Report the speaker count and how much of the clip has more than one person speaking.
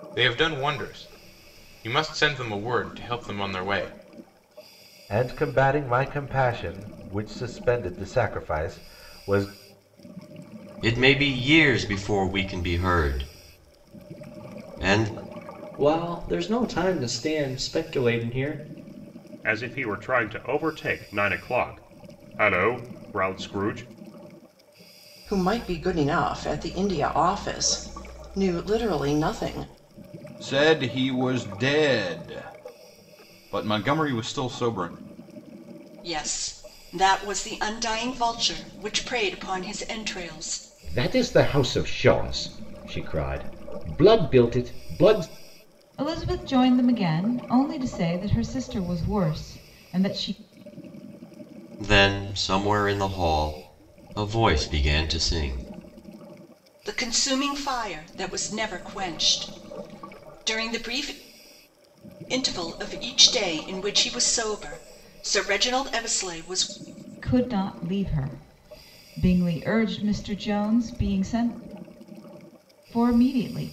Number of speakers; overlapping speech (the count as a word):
ten, no overlap